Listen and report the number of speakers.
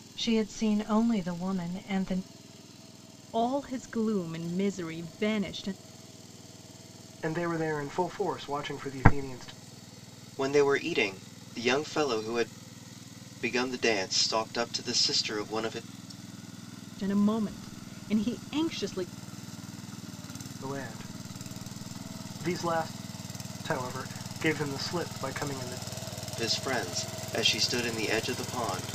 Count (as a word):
four